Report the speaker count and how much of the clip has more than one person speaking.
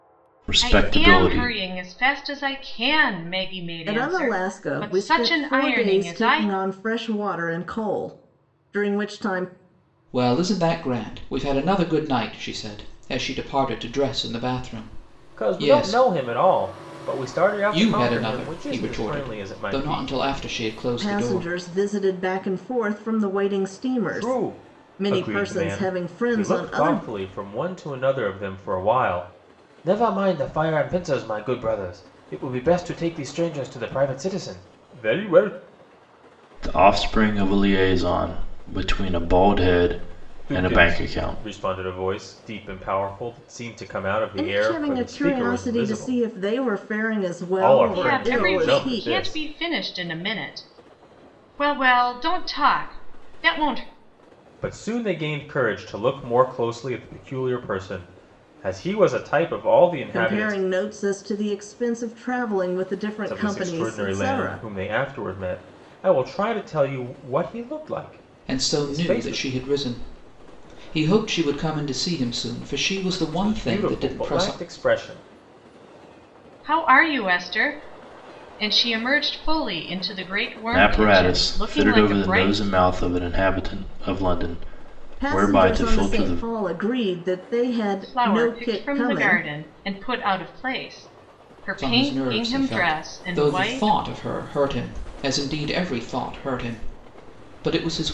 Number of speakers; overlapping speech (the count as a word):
five, about 27%